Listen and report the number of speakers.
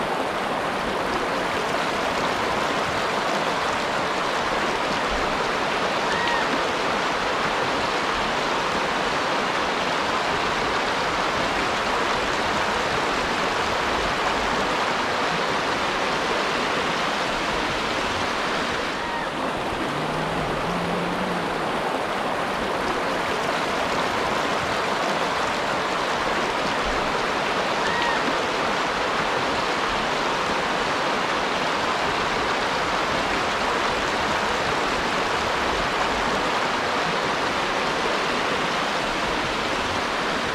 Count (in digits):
0